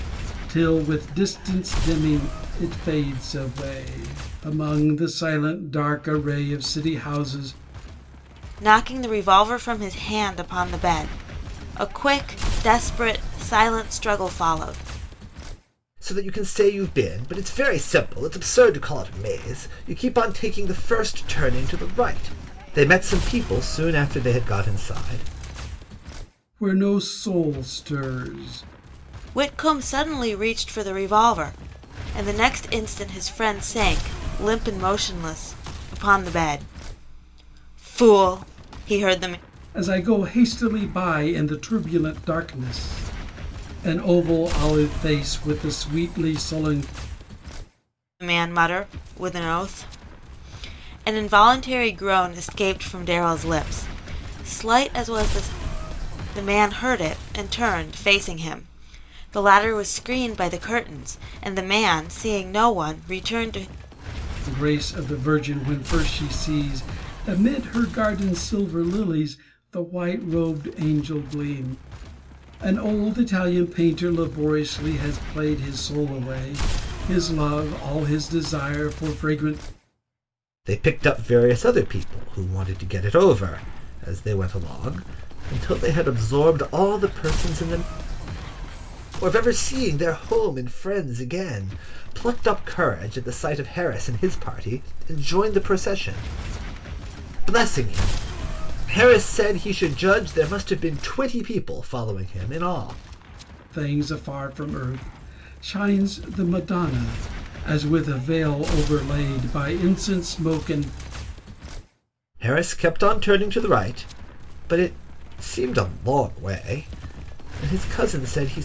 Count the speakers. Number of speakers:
three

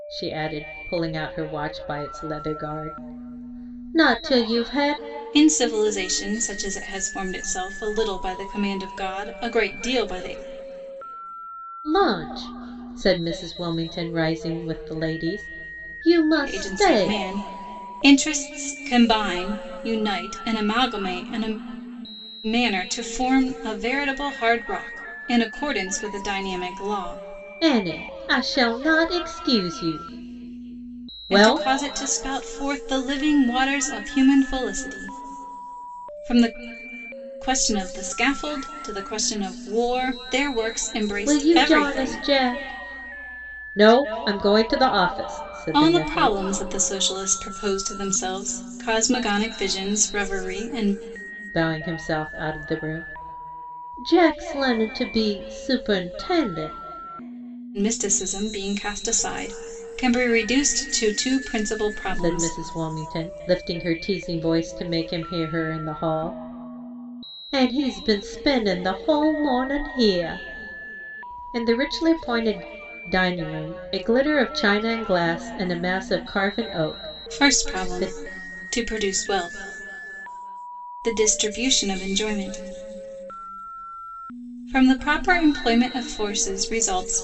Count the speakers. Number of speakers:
two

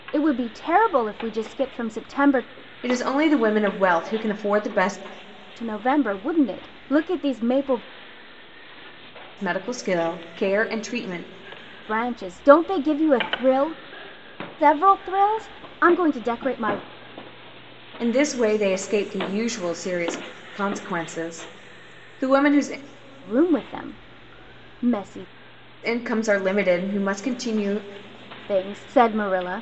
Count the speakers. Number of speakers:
two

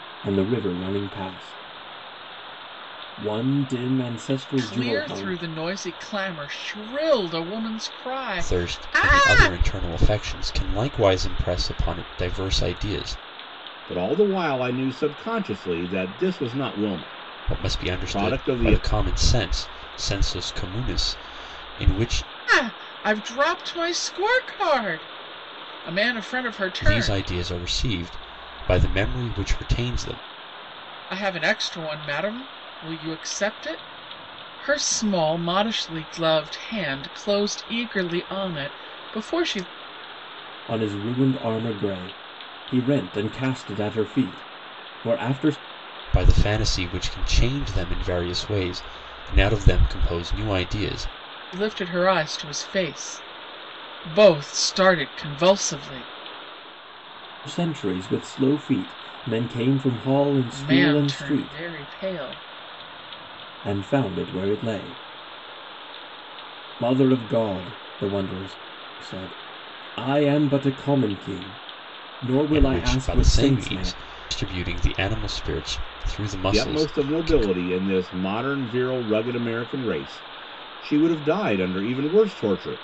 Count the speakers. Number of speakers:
four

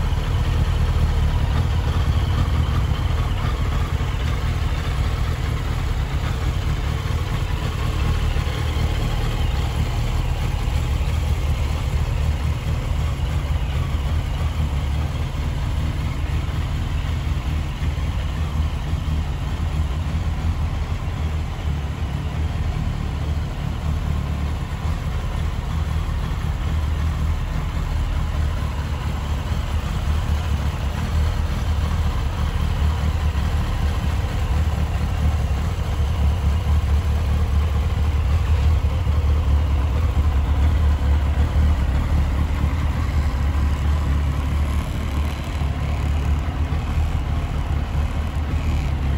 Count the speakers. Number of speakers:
zero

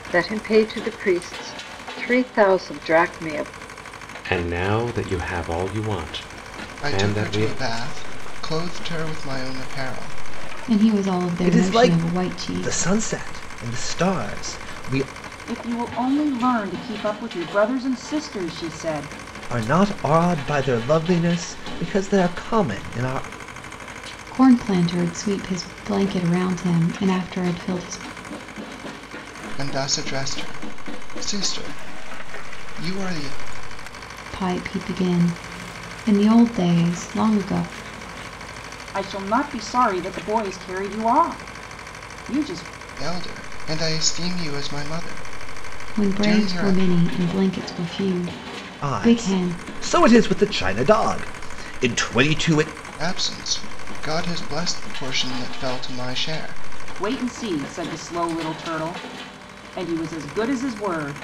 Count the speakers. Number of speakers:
six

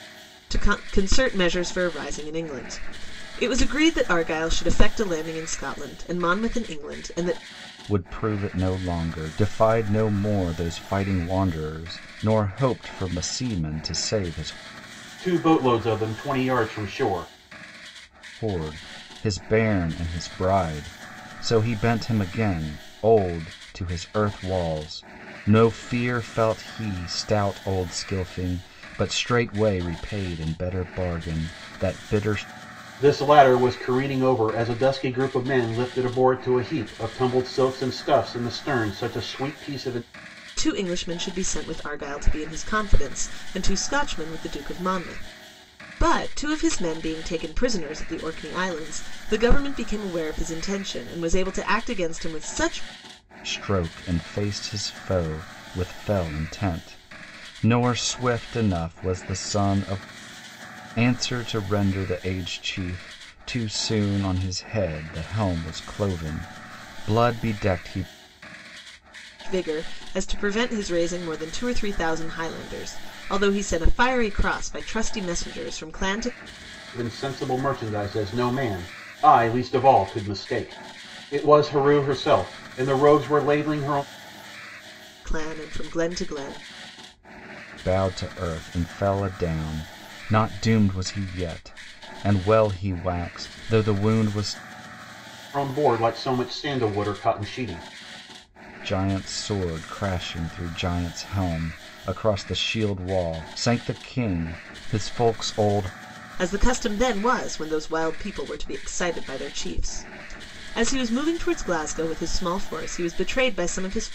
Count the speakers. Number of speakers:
three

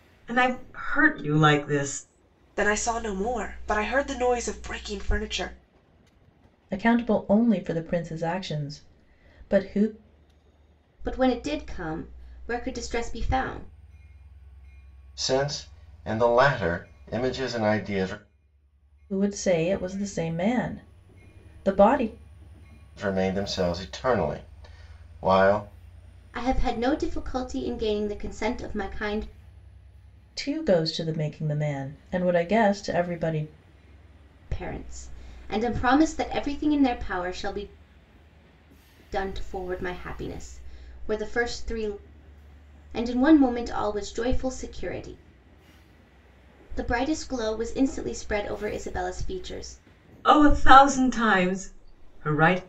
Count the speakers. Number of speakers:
five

